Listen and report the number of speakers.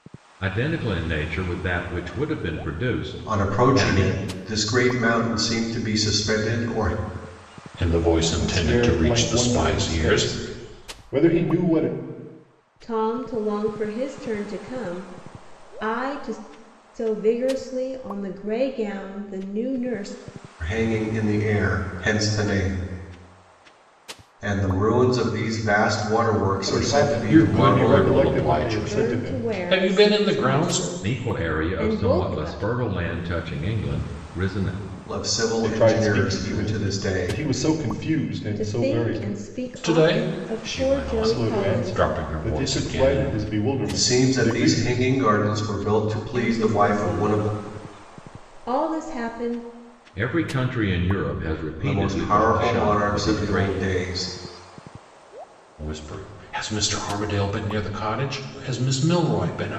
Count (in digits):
5